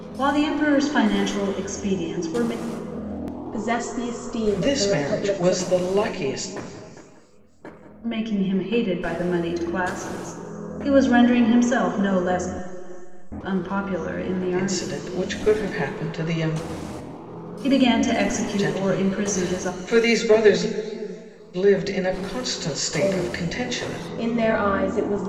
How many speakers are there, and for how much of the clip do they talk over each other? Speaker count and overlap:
3, about 15%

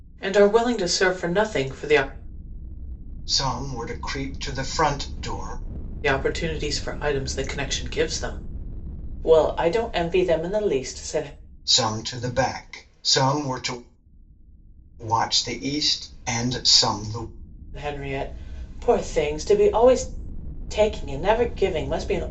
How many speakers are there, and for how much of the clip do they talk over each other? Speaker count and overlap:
2, no overlap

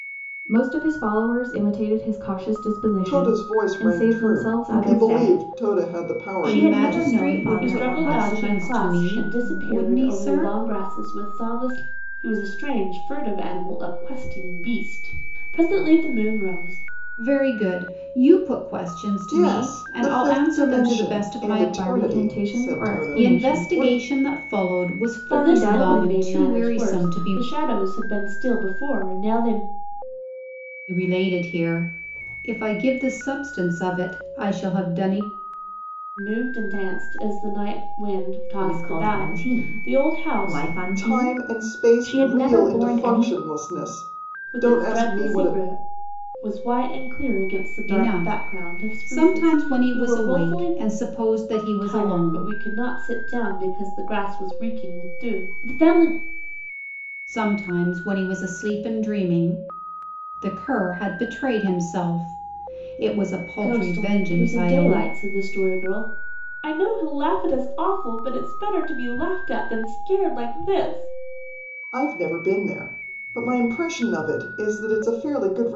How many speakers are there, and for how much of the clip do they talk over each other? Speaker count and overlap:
5, about 35%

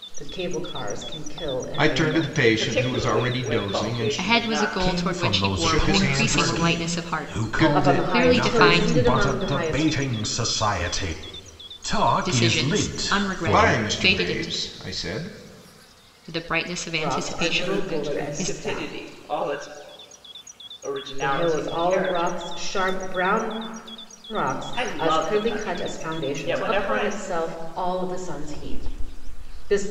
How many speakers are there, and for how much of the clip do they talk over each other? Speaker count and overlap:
5, about 54%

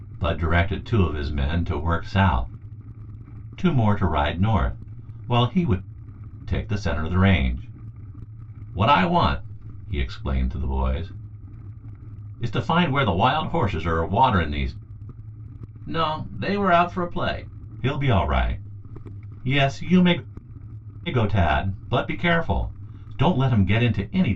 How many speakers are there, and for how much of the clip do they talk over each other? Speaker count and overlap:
1, no overlap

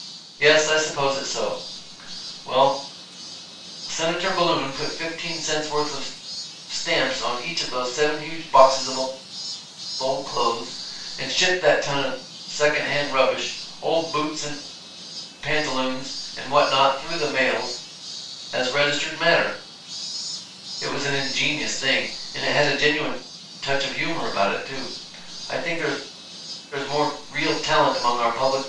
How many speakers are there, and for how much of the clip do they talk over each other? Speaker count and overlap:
1, no overlap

